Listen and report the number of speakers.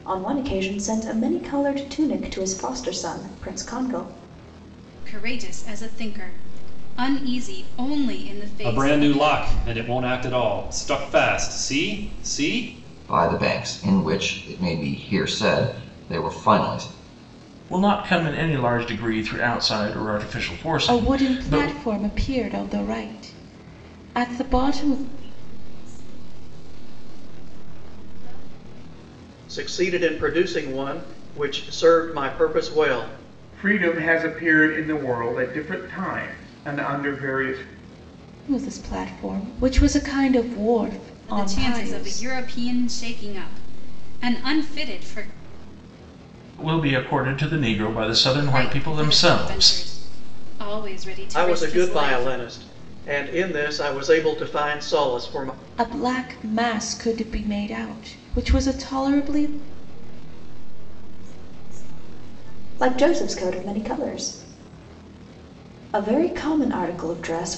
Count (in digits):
9